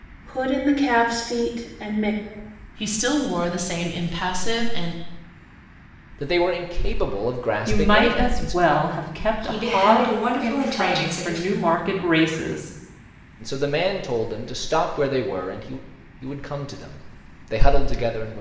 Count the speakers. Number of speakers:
5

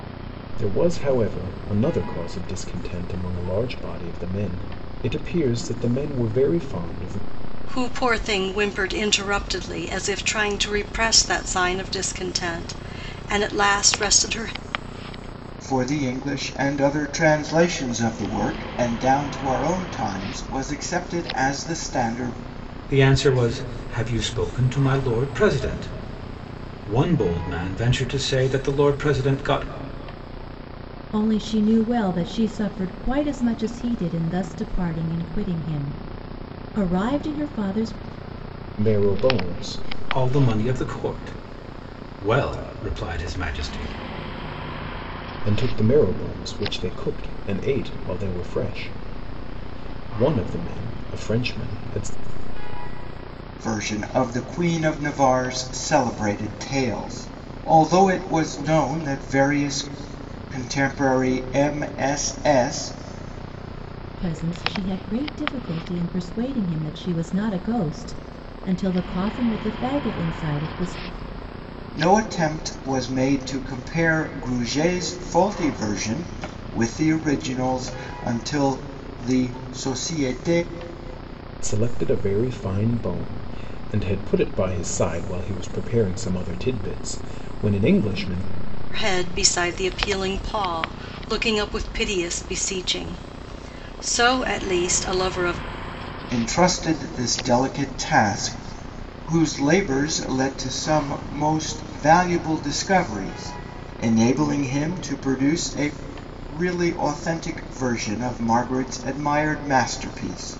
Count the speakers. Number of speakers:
5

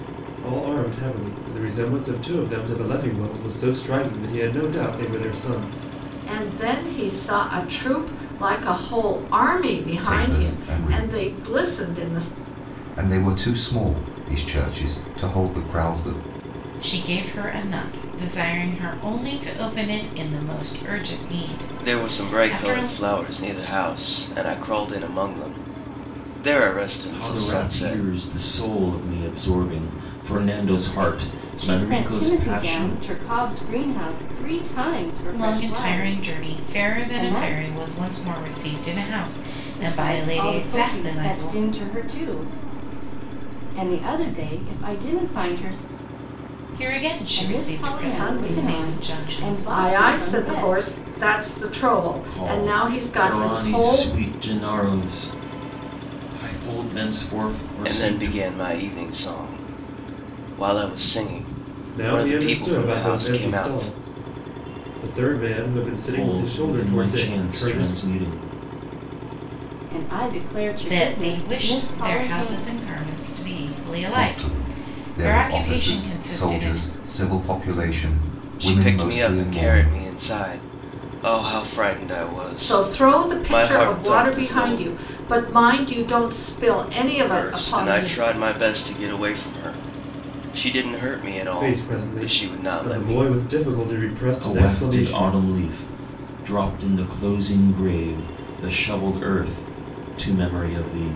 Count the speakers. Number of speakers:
7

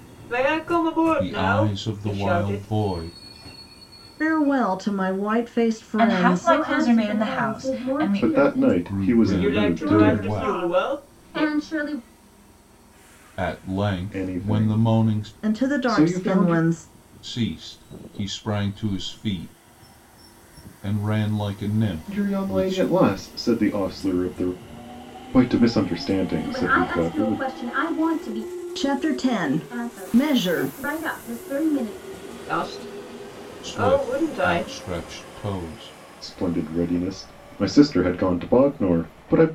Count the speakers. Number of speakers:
6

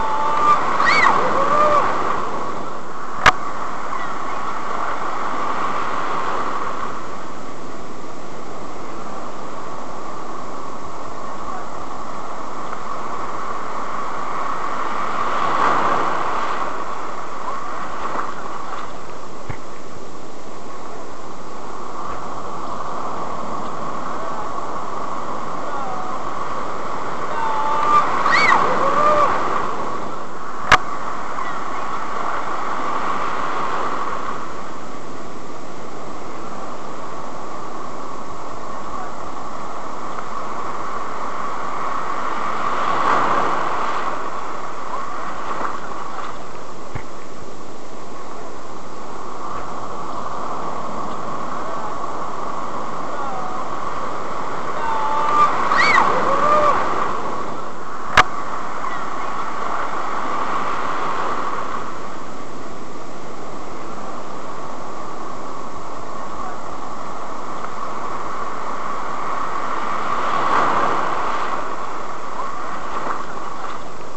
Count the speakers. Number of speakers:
0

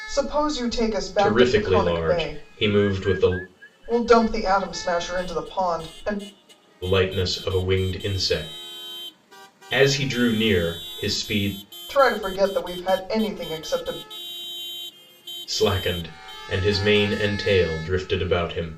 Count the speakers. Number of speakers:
2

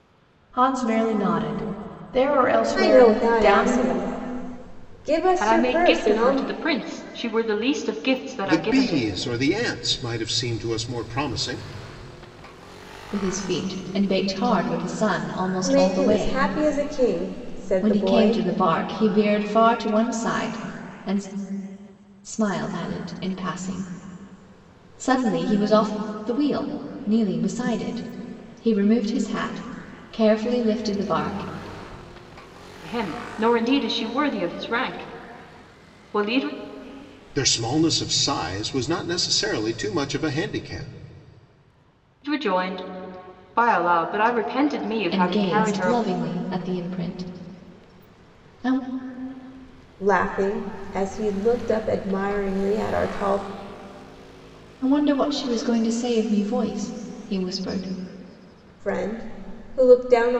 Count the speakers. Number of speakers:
5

